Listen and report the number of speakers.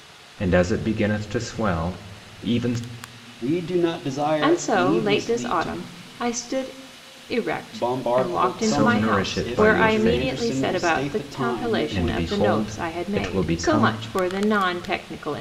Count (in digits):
3